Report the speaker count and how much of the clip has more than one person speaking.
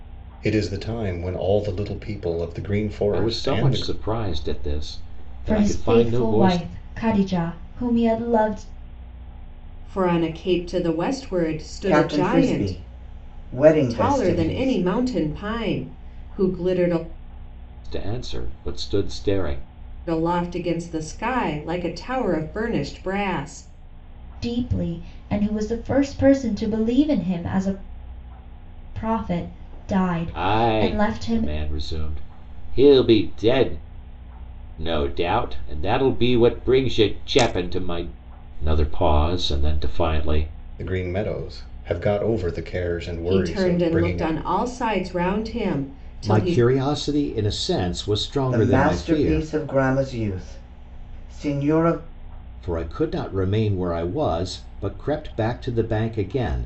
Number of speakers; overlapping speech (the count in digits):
5, about 14%